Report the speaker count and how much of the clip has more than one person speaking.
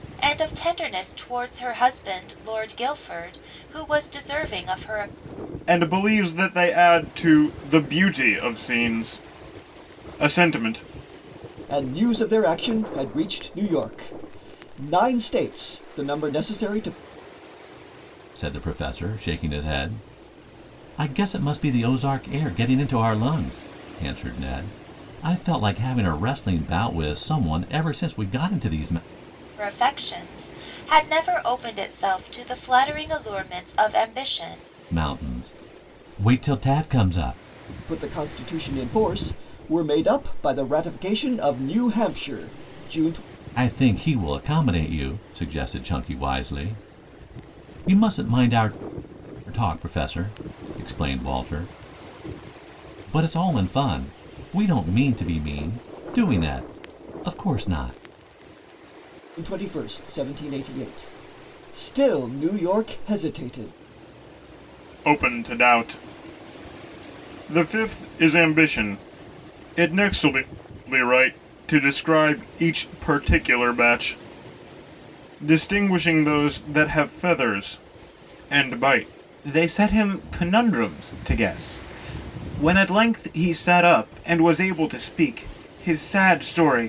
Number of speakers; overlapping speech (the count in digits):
4, no overlap